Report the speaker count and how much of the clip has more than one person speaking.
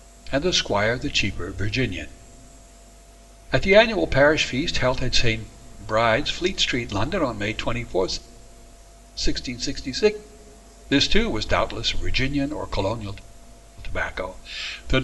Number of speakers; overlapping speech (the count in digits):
1, no overlap